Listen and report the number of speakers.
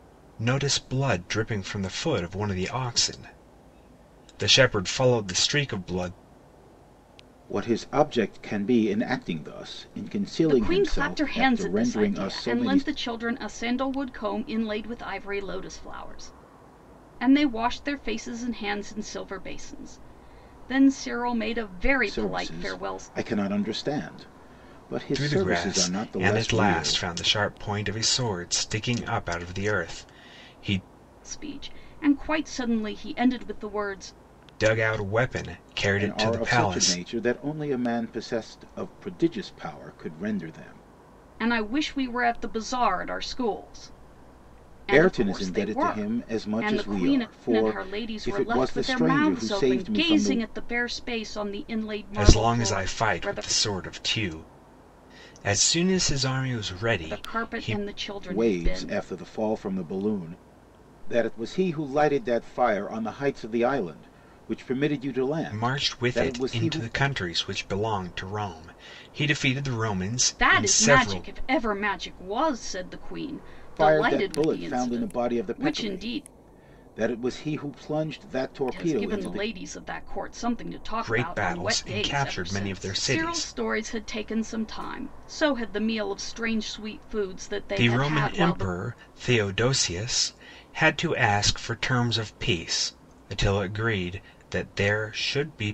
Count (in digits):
3